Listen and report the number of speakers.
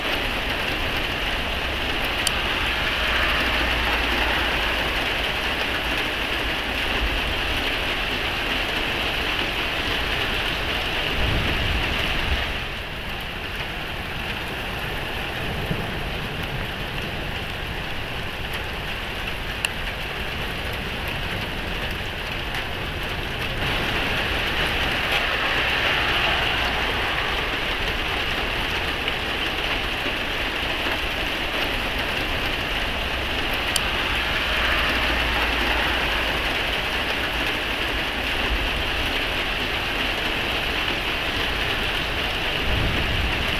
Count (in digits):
0